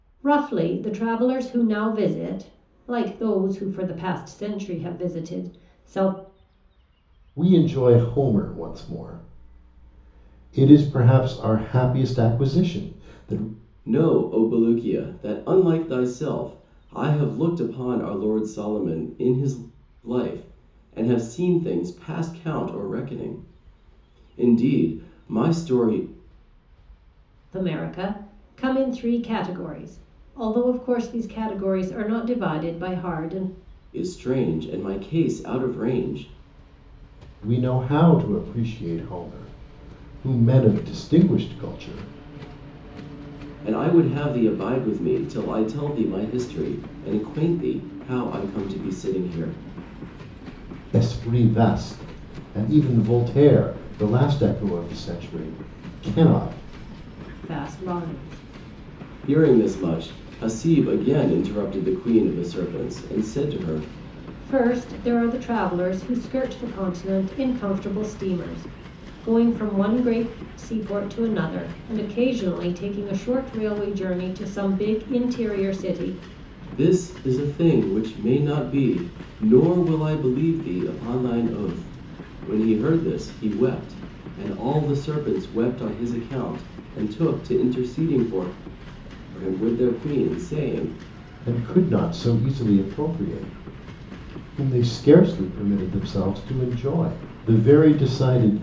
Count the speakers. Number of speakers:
3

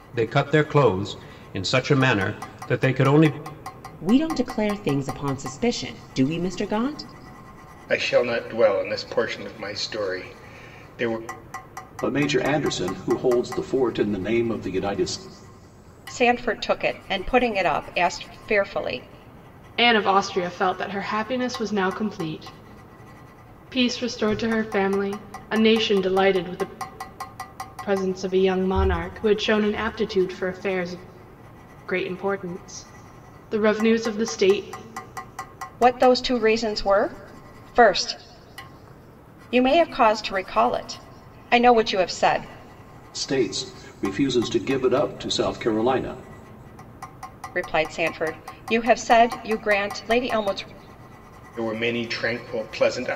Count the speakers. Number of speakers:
6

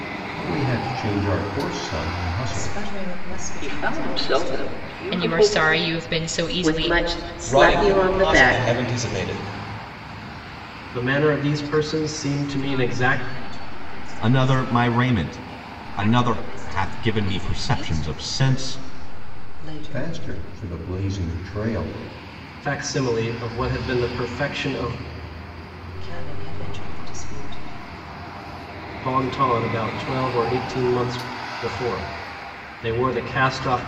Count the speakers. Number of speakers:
9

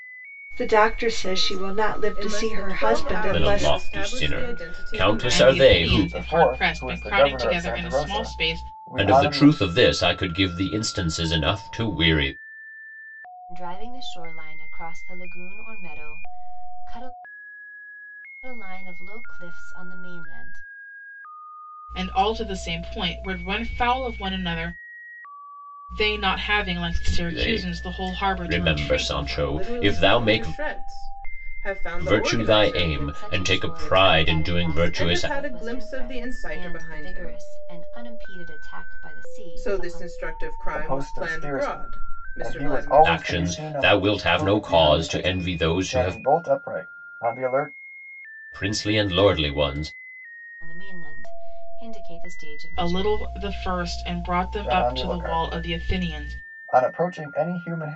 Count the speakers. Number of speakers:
6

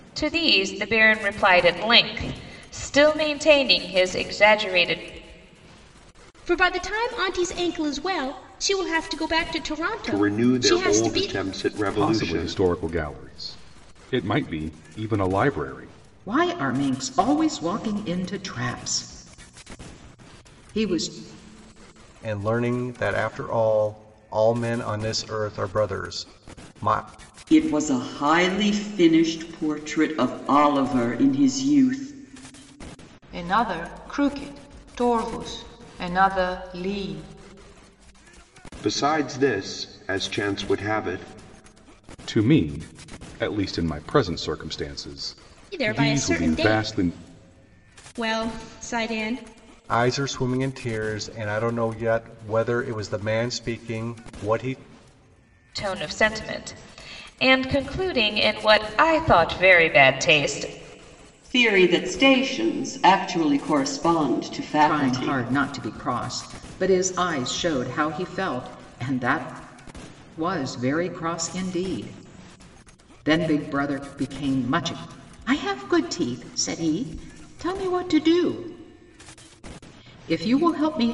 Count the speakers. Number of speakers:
8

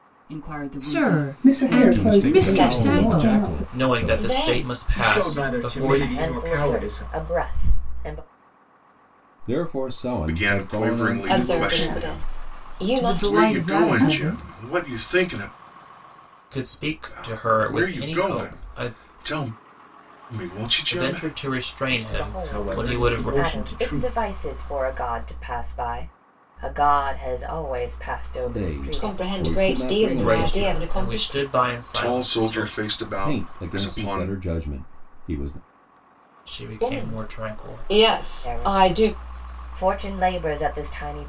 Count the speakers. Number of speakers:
10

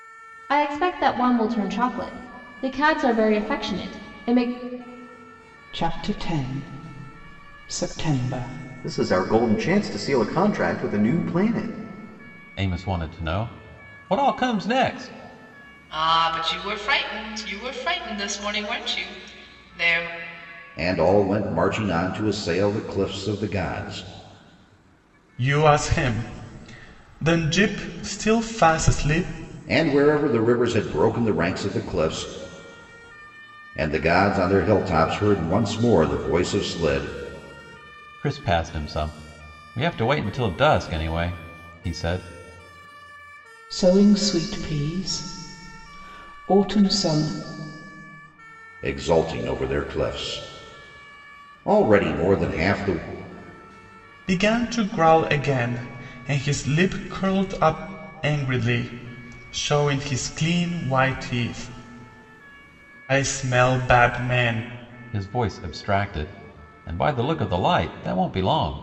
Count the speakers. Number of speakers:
7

